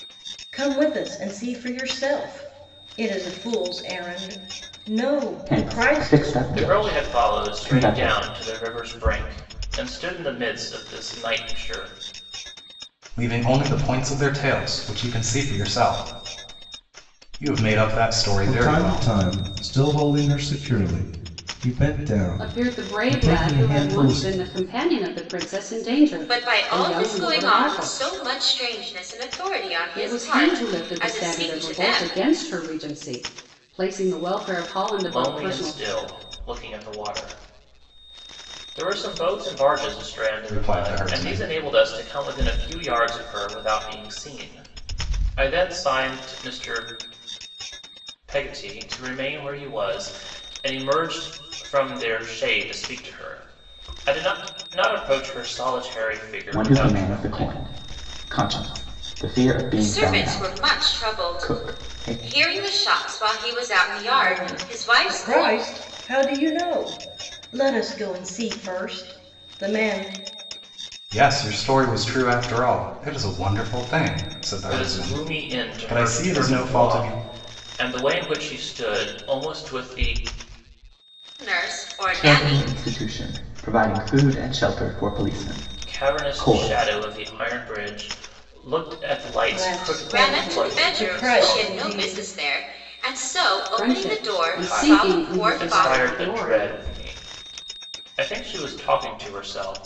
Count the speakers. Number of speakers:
seven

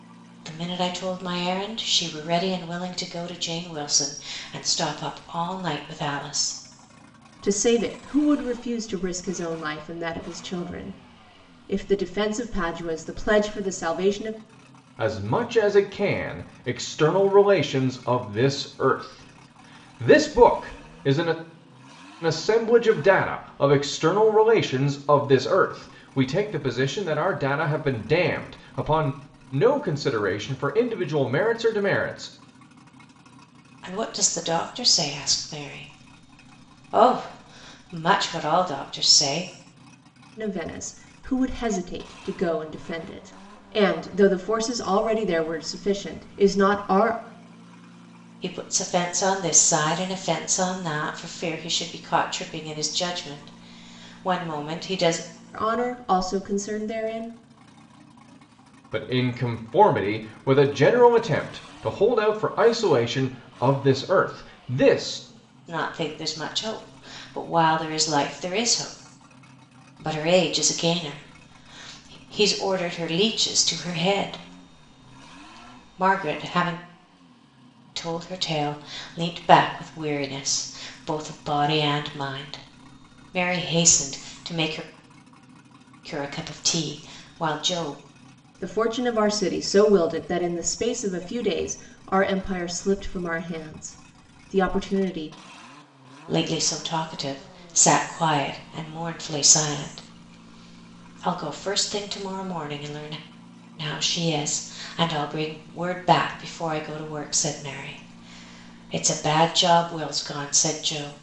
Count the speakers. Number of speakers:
three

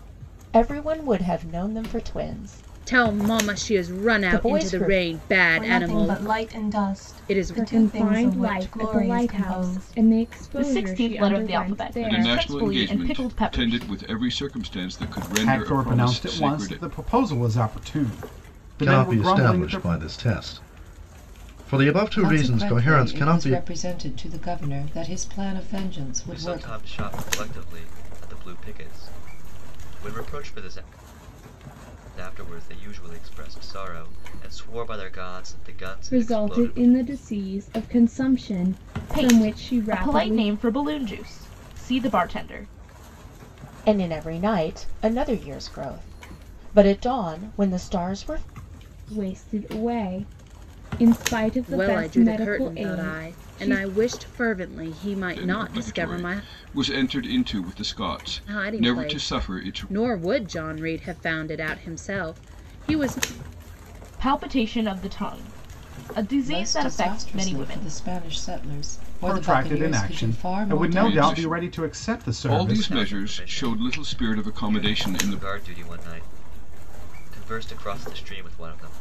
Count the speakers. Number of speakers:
ten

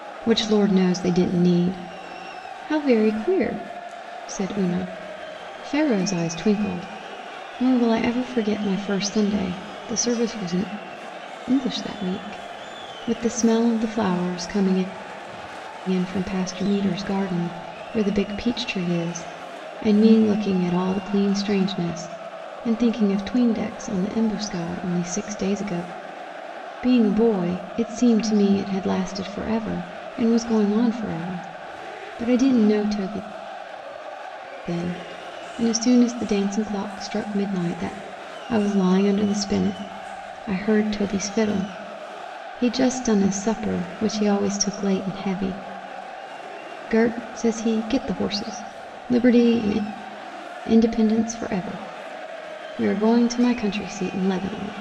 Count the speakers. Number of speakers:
one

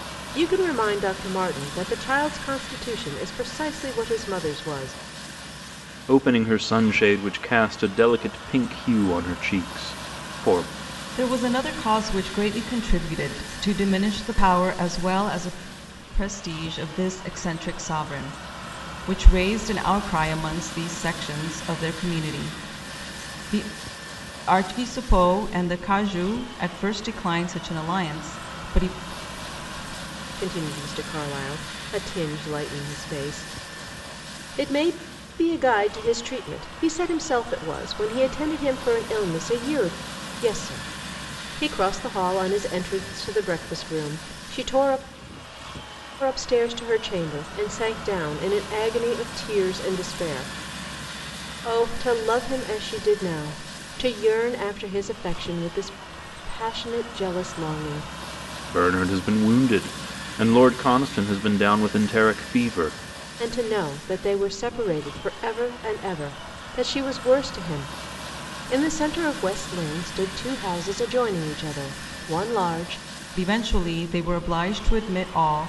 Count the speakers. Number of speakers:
three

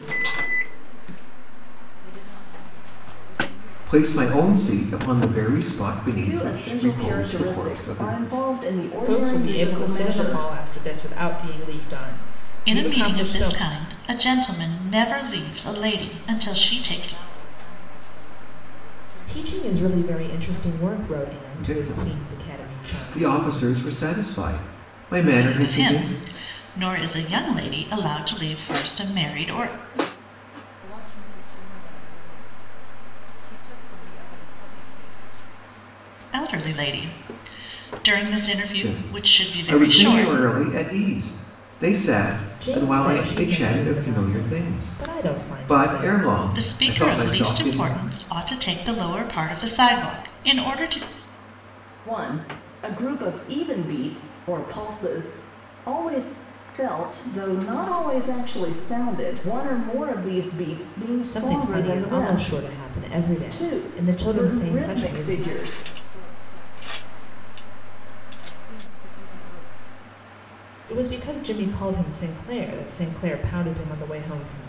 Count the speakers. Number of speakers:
five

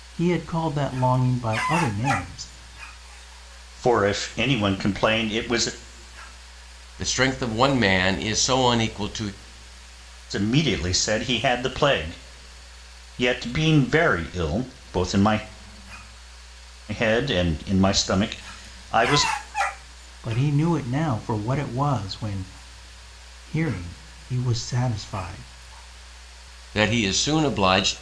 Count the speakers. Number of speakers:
three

